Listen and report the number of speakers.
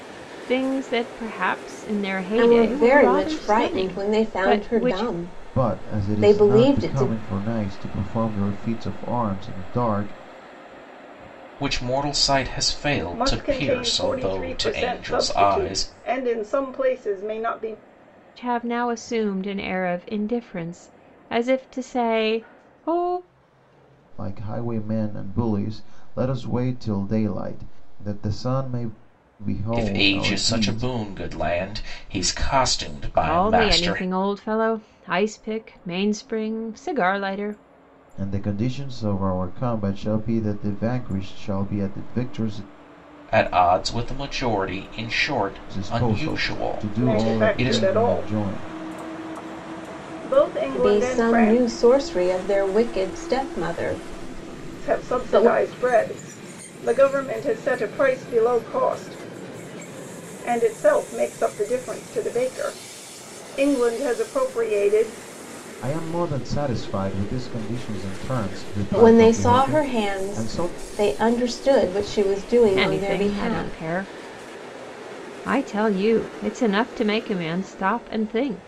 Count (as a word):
five